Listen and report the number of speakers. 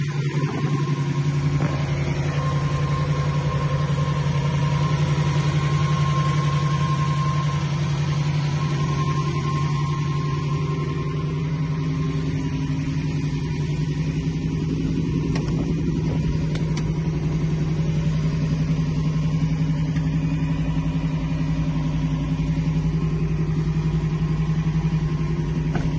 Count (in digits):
0